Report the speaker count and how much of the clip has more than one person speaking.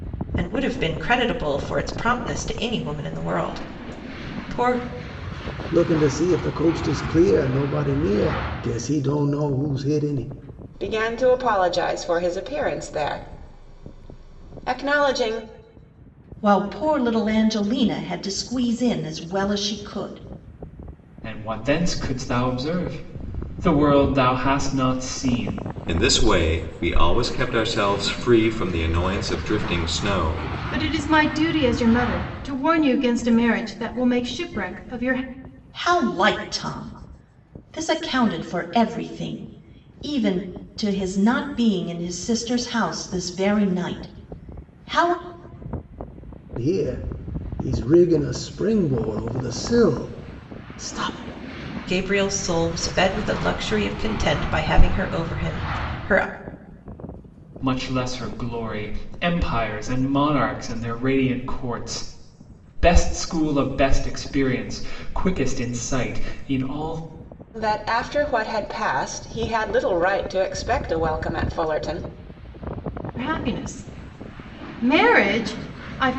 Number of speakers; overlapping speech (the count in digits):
7, no overlap